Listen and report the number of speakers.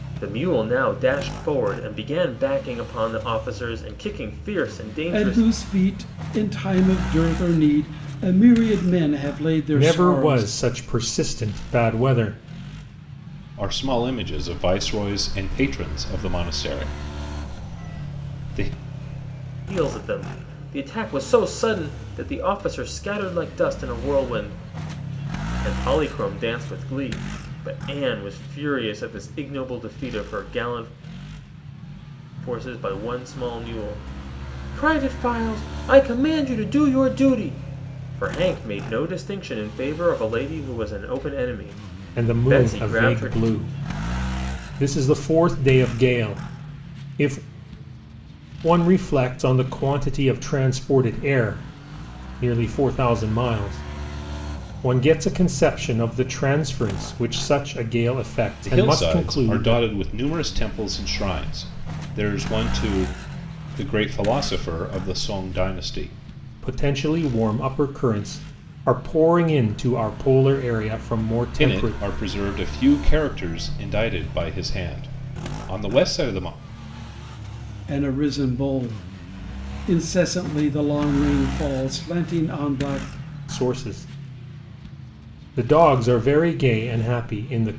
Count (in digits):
4